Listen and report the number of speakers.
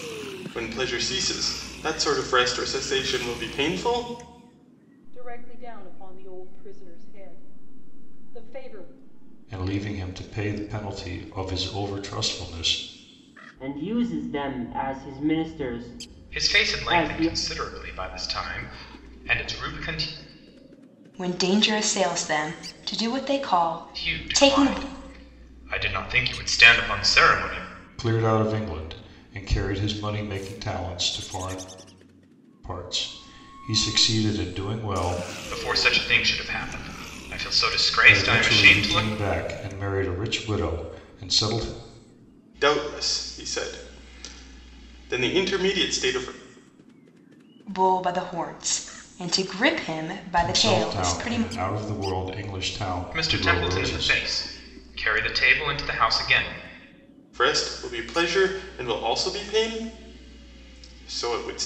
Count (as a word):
six